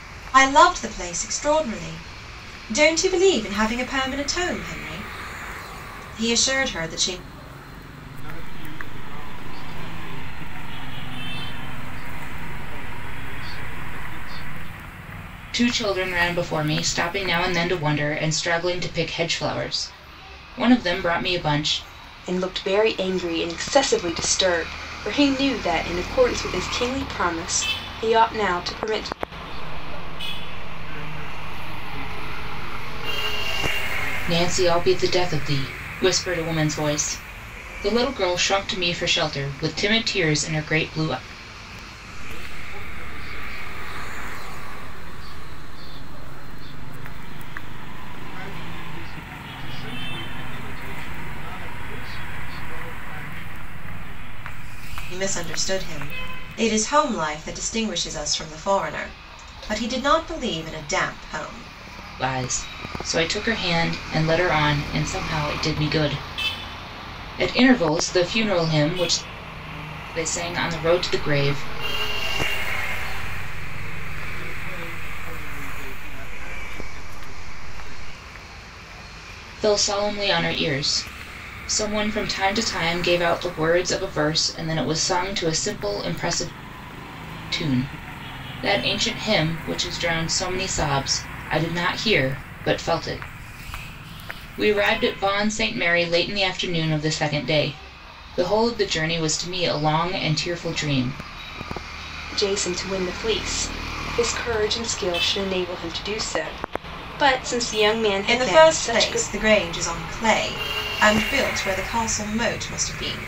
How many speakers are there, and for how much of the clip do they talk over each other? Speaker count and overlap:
four, about 4%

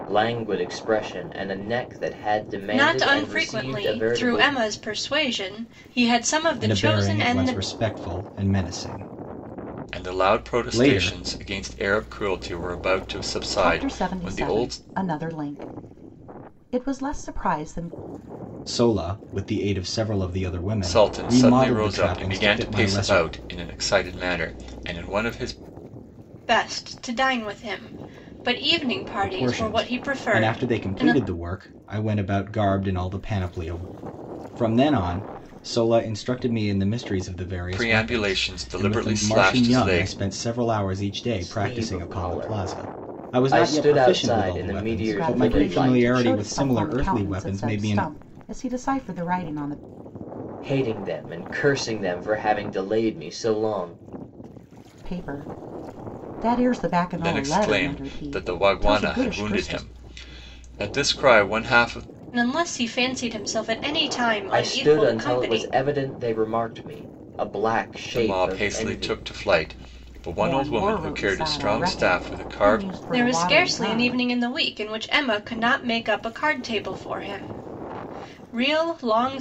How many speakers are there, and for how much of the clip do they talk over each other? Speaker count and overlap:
five, about 35%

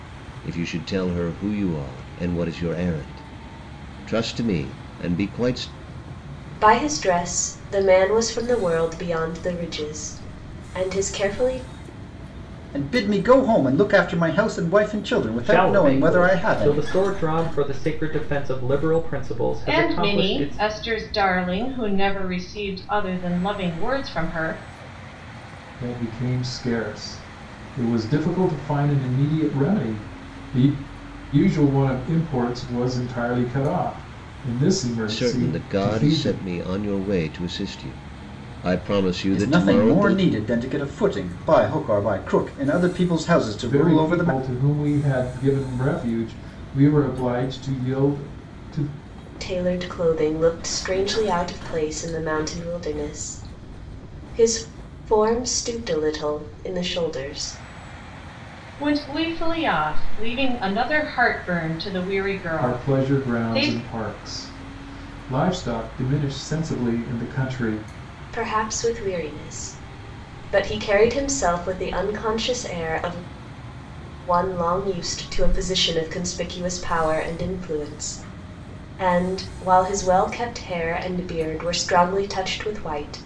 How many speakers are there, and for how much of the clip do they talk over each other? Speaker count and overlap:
six, about 8%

